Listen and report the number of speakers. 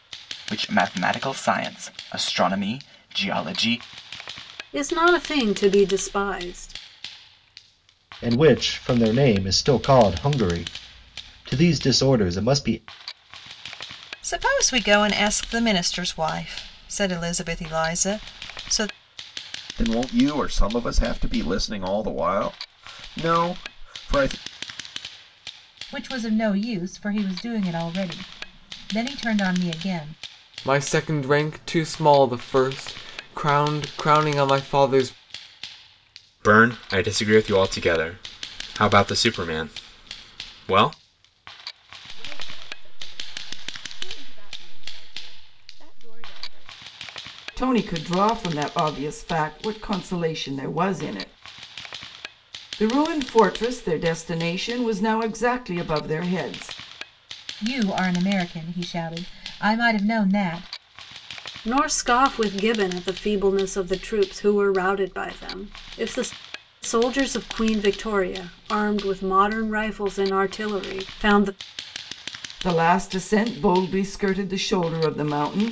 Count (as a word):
ten